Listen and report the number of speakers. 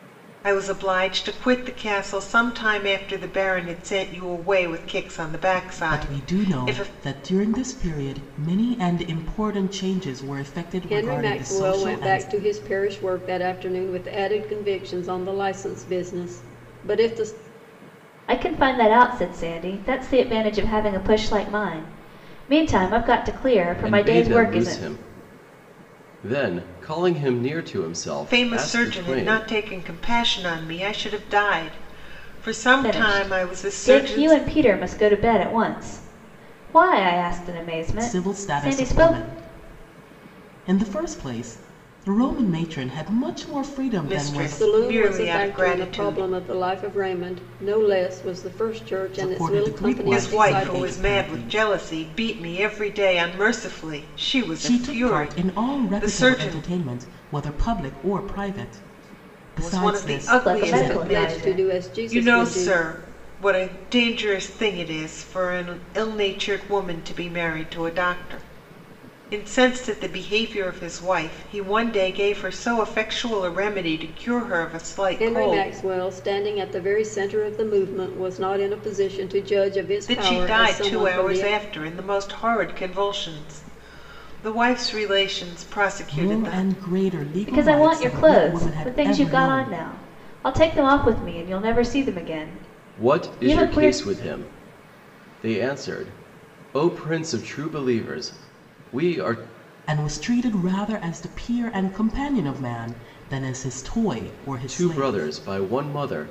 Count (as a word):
five